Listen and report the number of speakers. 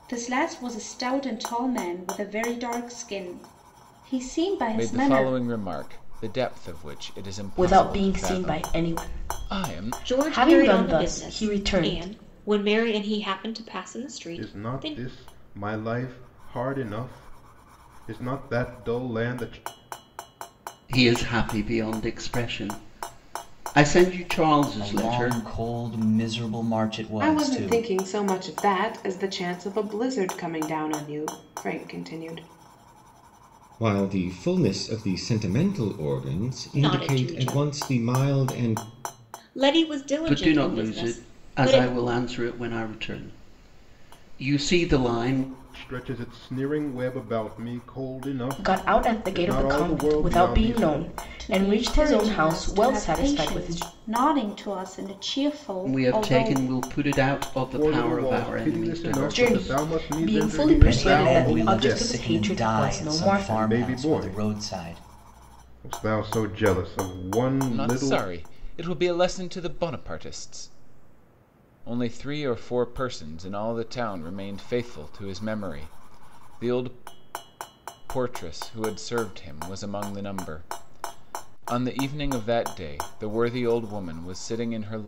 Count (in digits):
9